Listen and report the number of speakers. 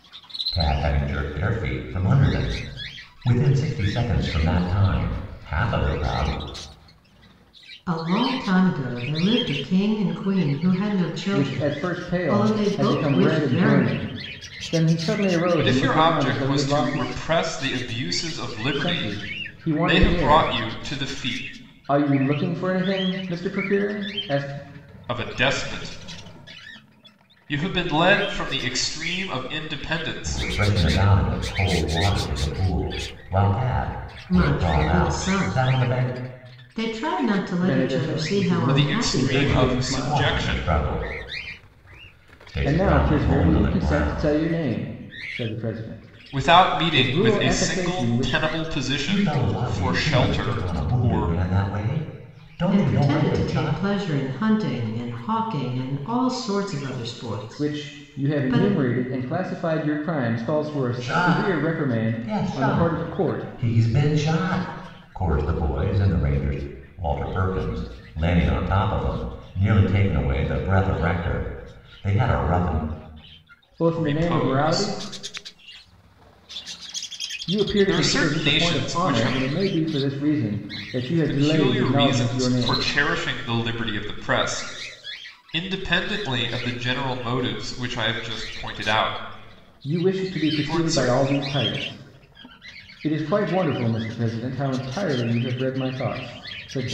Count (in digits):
4